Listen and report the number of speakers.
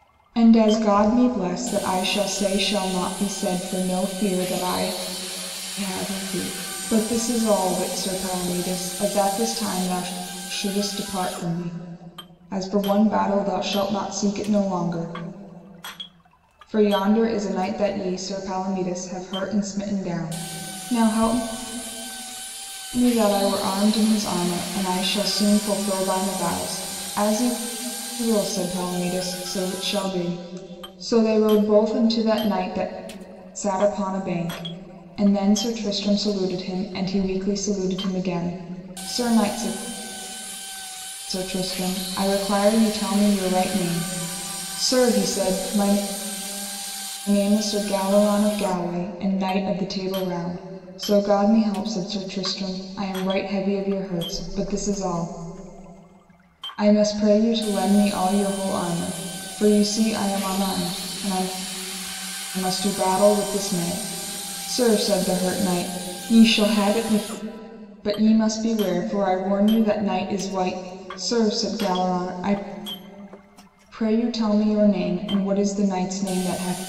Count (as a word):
one